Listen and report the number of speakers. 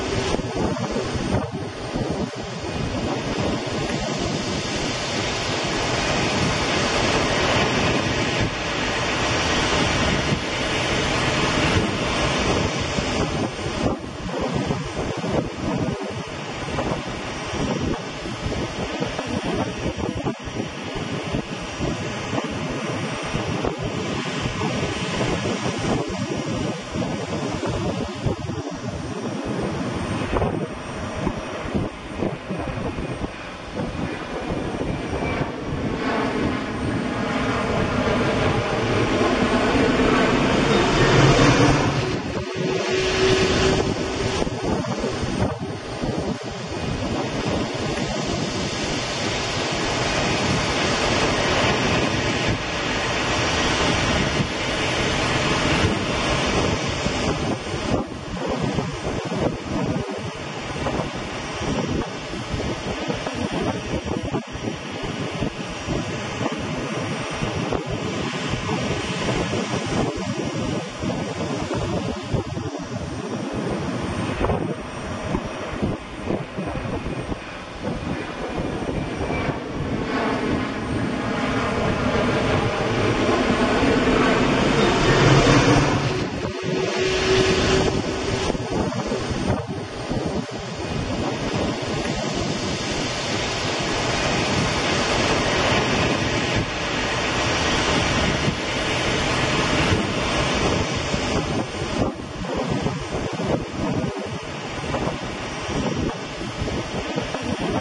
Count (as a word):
zero